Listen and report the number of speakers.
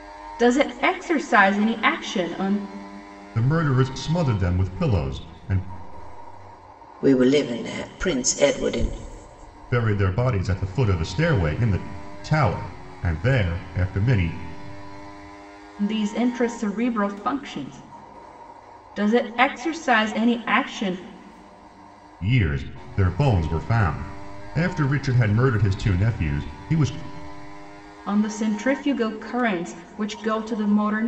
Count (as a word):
three